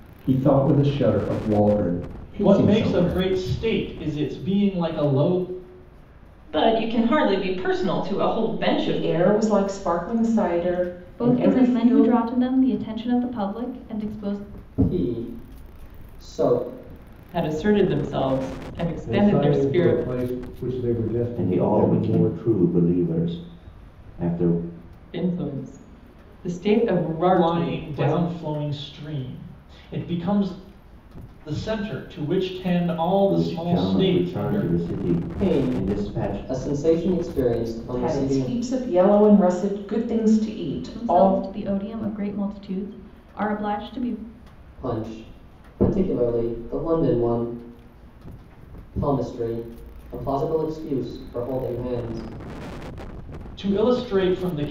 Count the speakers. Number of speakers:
9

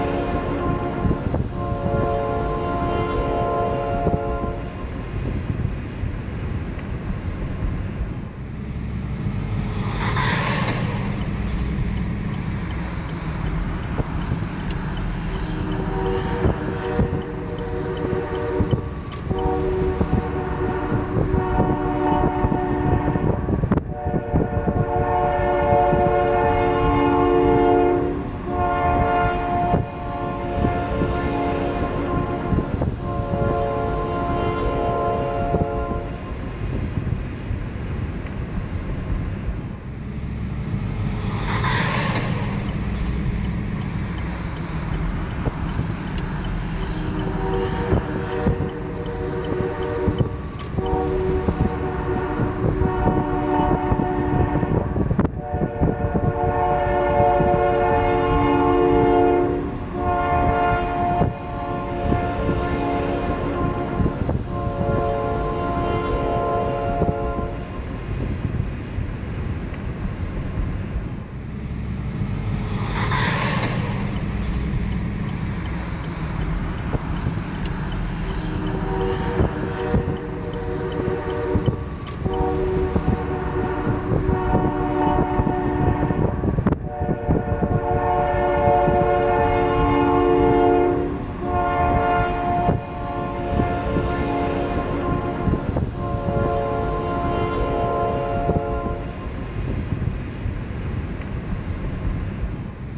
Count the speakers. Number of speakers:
0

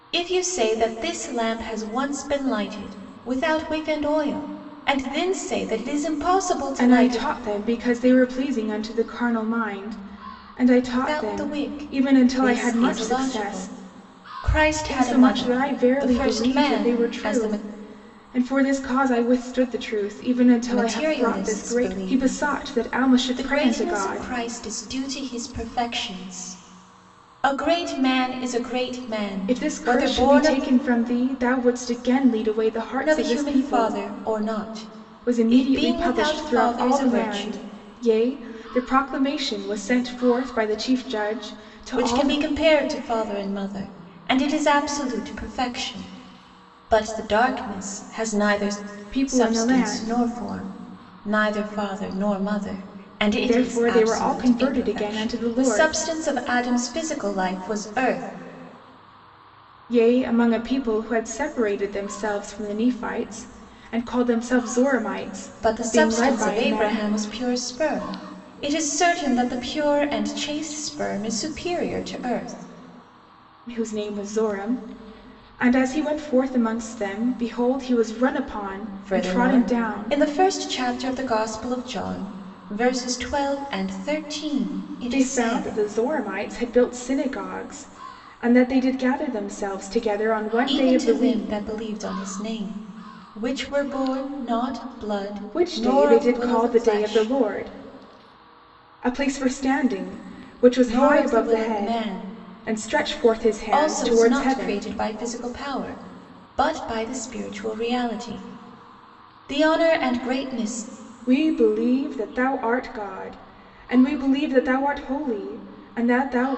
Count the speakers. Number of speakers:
2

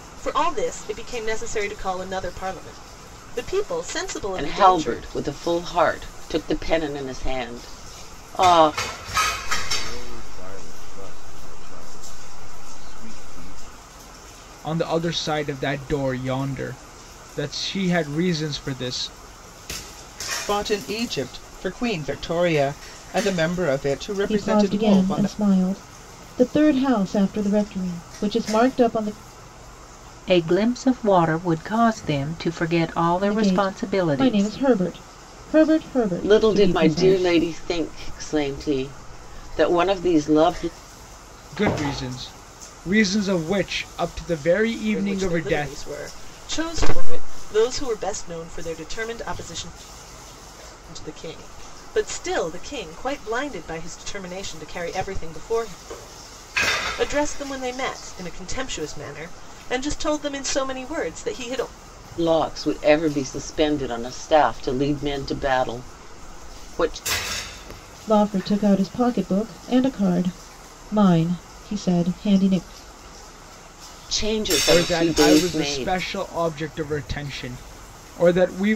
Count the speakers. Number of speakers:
7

